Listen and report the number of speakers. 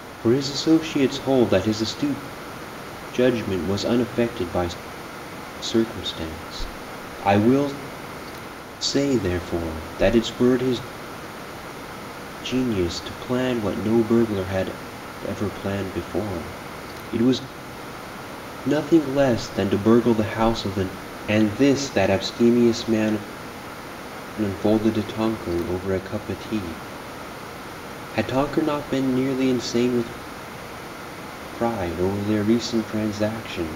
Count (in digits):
1